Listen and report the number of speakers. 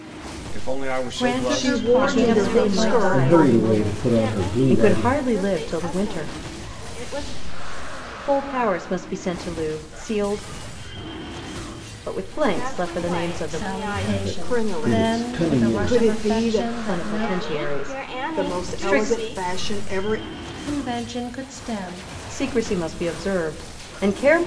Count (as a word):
six